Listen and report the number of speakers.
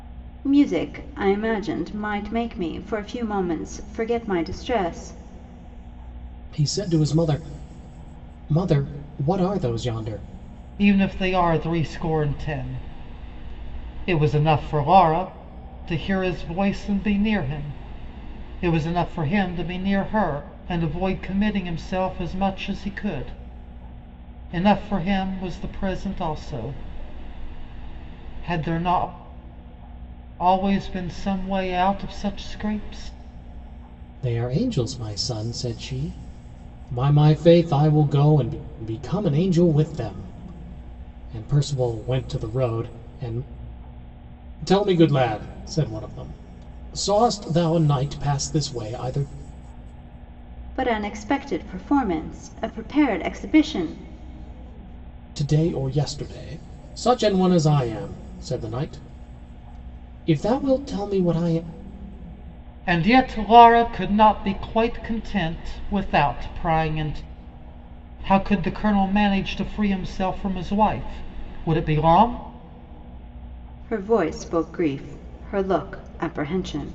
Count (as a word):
three